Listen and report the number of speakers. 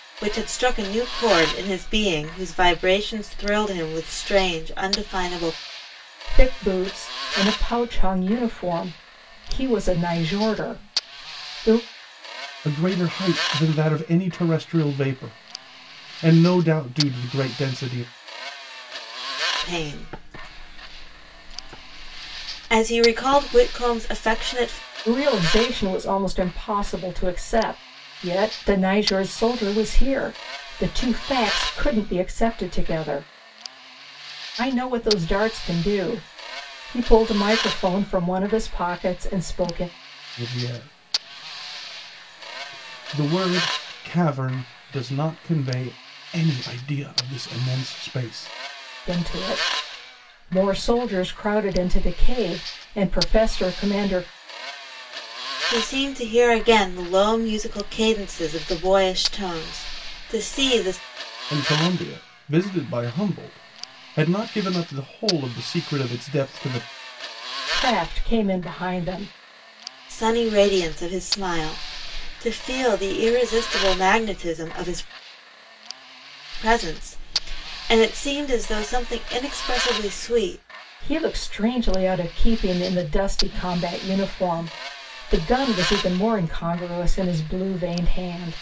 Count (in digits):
3